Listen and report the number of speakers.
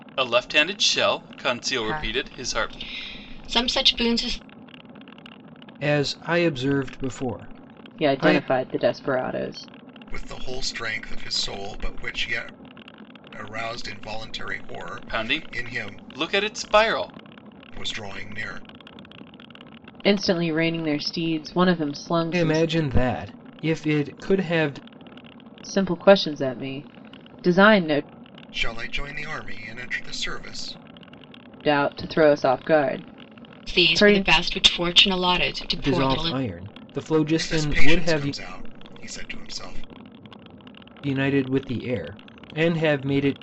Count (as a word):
five